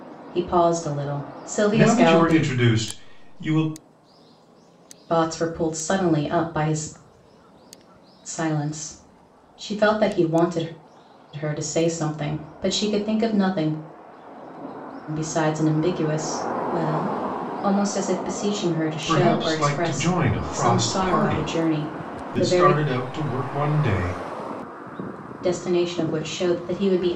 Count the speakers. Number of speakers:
2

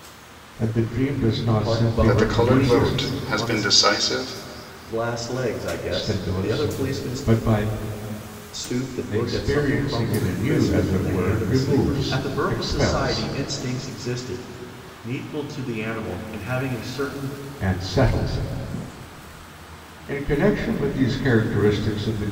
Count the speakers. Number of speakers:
3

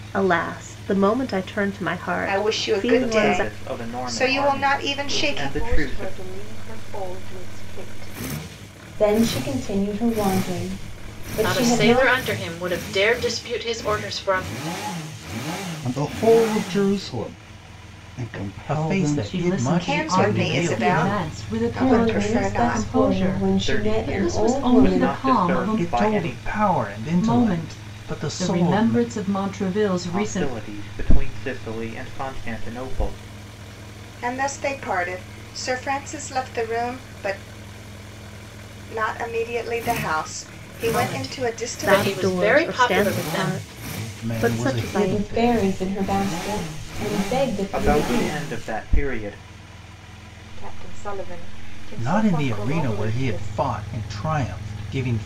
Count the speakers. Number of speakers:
9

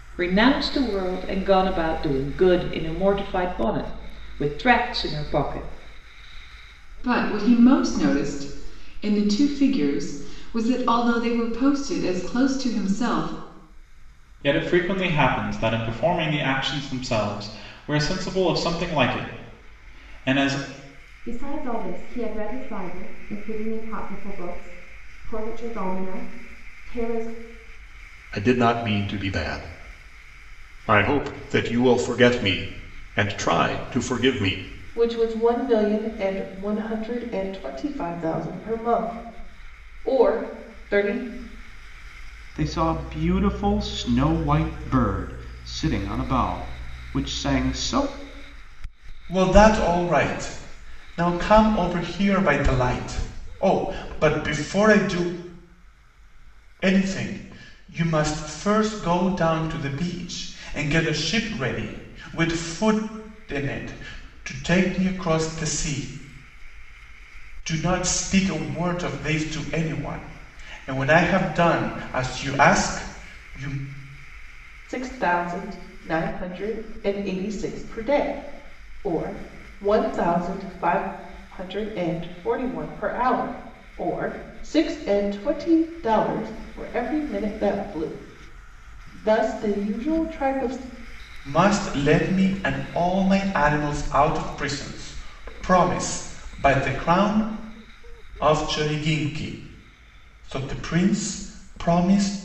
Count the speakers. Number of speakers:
8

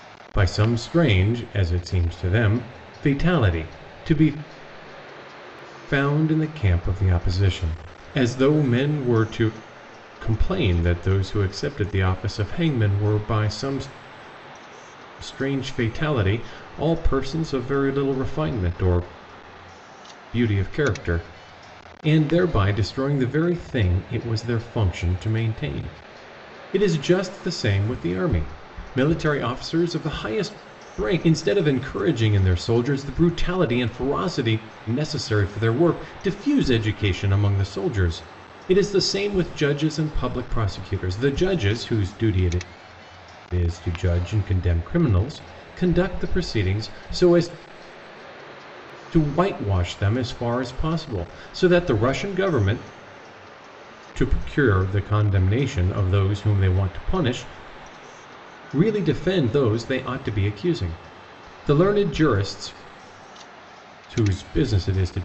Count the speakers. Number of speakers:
1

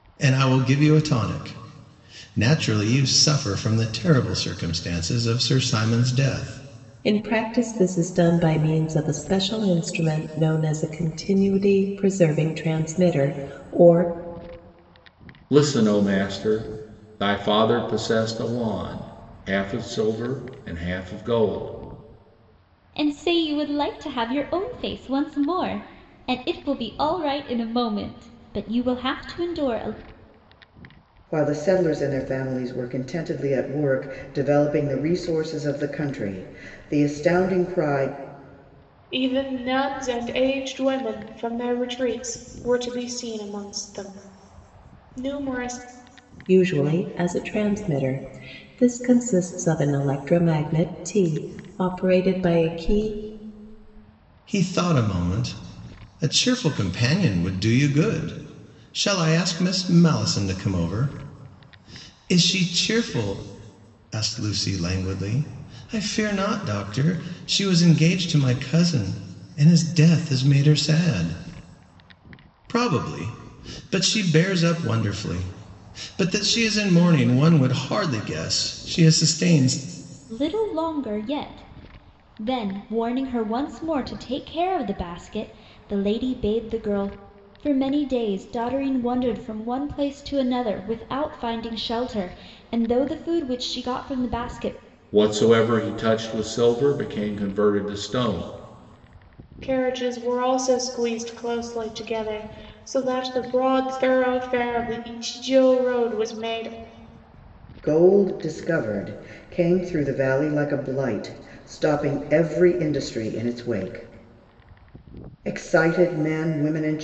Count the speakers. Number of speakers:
6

